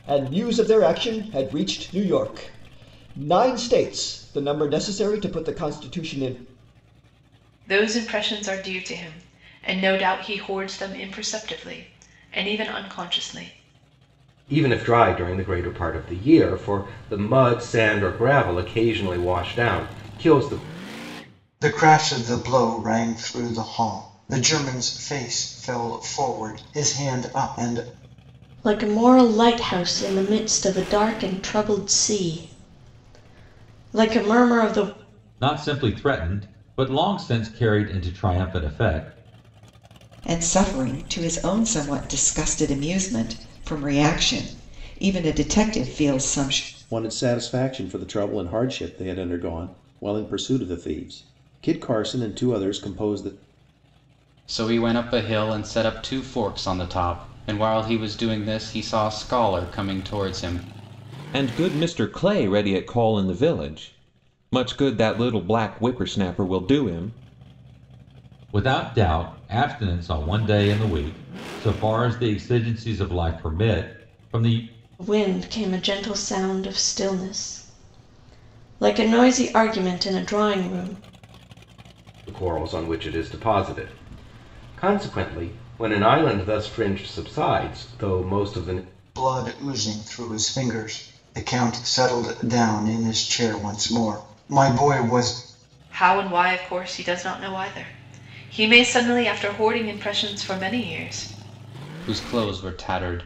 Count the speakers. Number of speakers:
ten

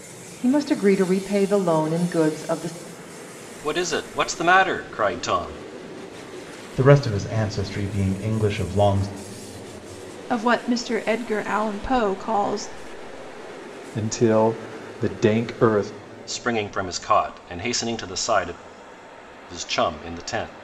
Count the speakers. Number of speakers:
five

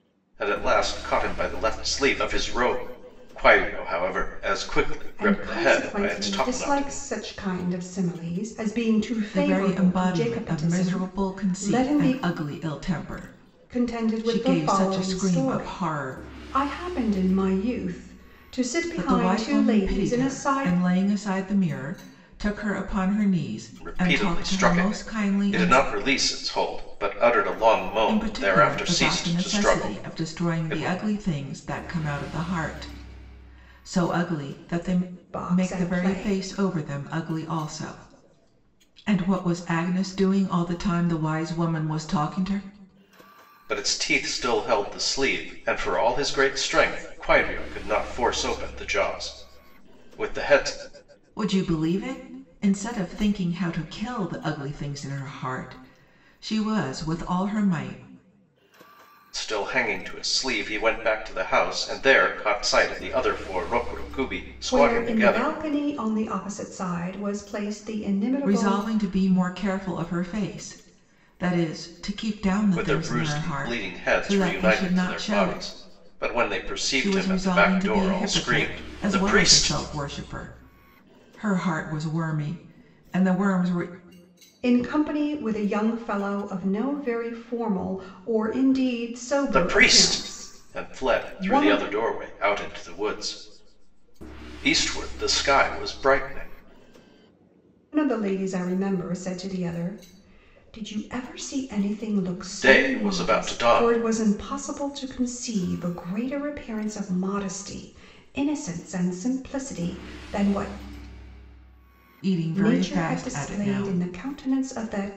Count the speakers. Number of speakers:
three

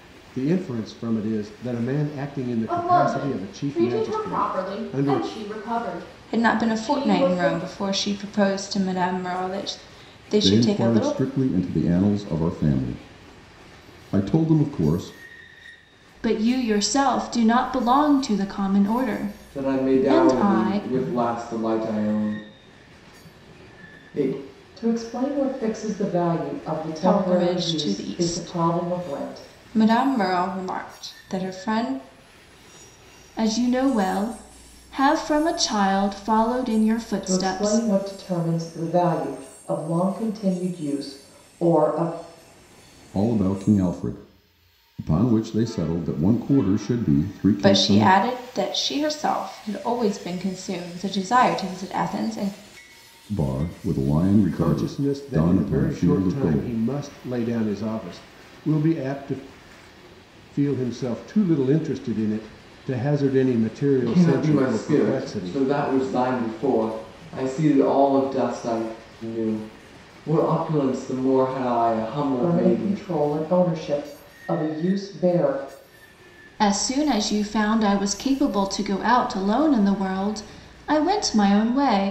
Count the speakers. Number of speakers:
seven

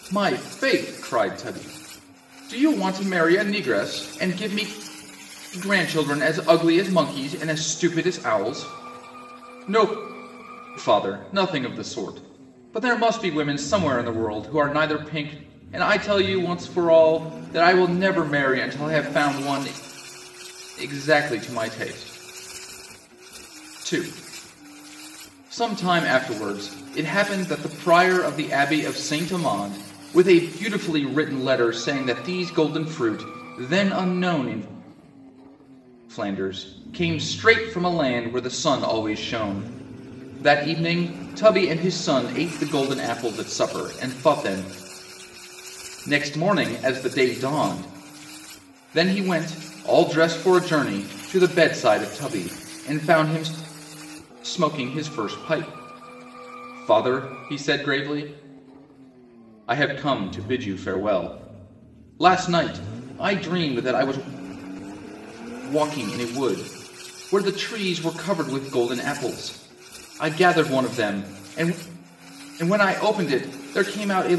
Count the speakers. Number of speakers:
one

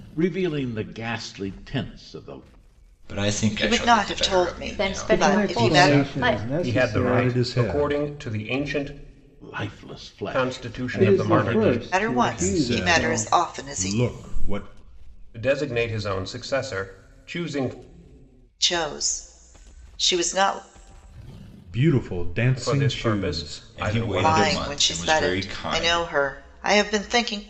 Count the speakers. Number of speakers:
seven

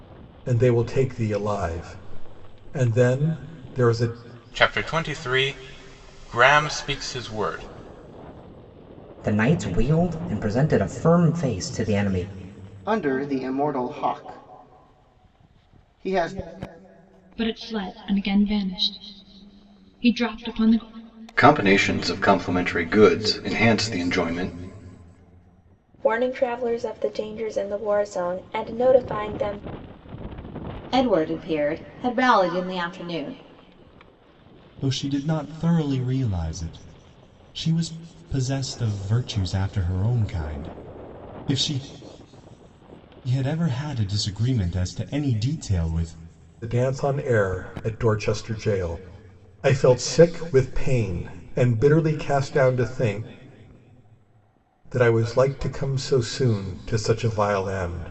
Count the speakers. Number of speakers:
nine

